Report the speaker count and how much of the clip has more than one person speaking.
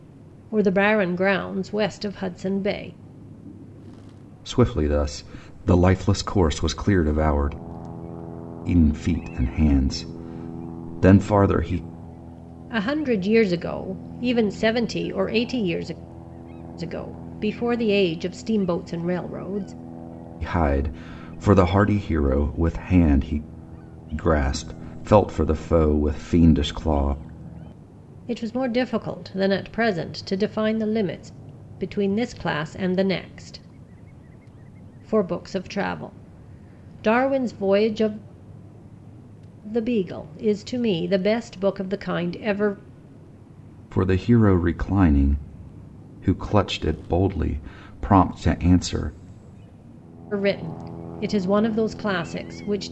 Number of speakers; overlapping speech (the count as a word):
two, no overlap